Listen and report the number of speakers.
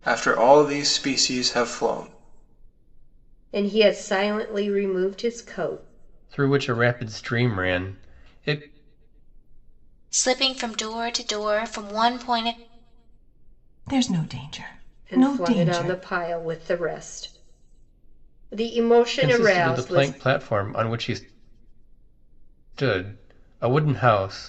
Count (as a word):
five